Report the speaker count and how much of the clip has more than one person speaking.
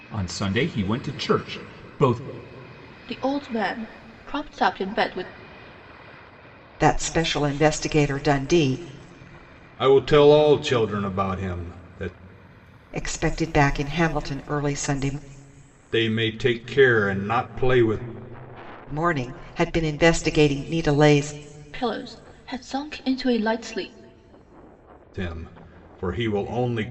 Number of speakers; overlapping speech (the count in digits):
4, no overlap